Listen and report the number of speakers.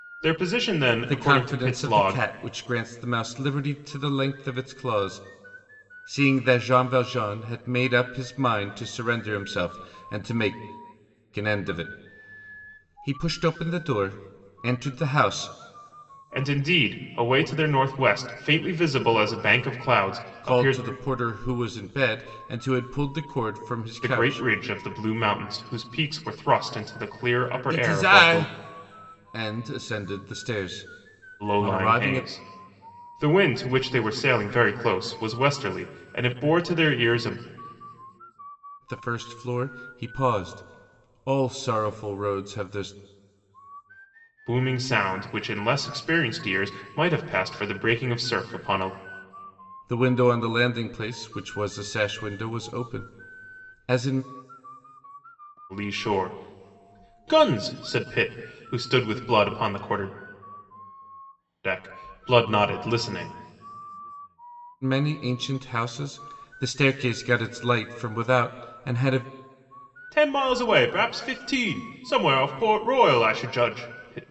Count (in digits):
2